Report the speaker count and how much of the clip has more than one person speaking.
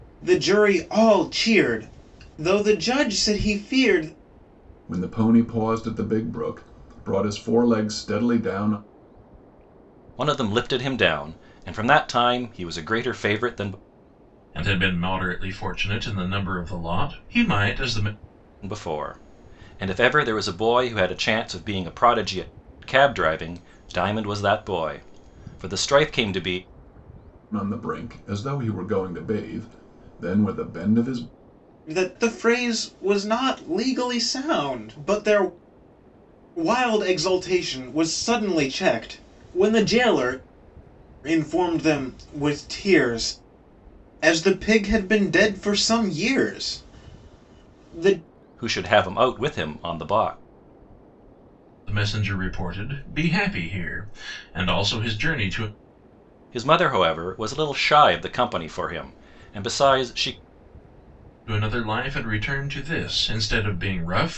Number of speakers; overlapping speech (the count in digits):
4, no overlap